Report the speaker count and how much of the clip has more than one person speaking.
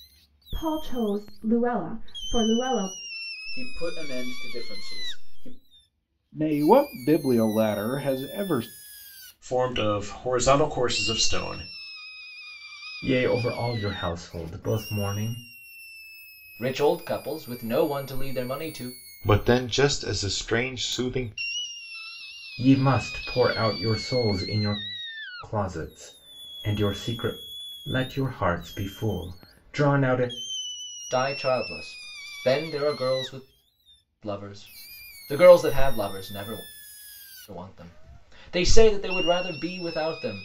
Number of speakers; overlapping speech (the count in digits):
7, no overlap